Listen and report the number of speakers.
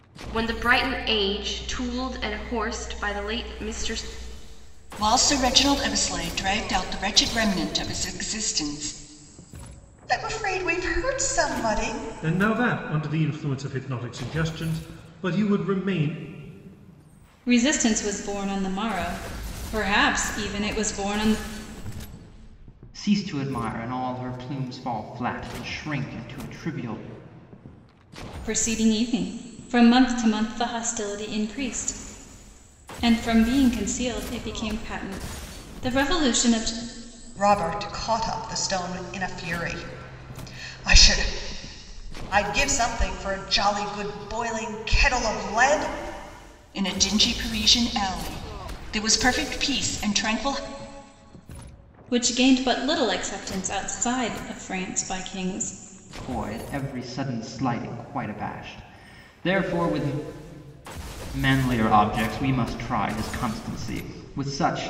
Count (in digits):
6